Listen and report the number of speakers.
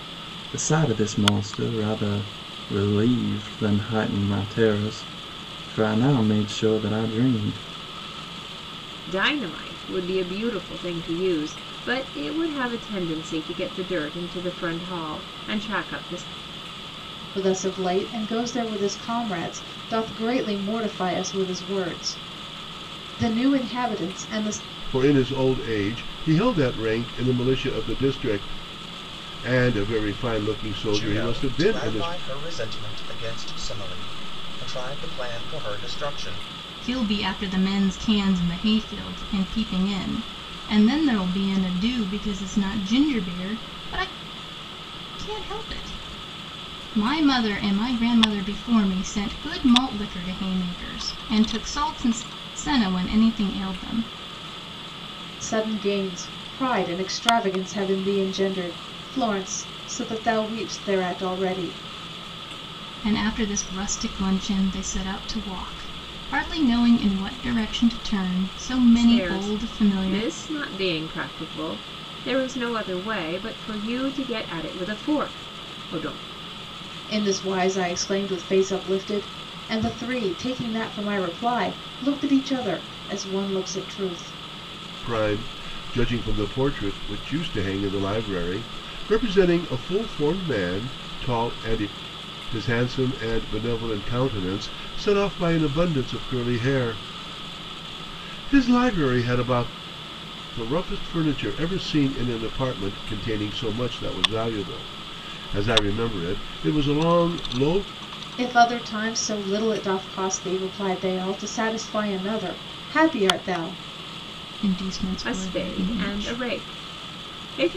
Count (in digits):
6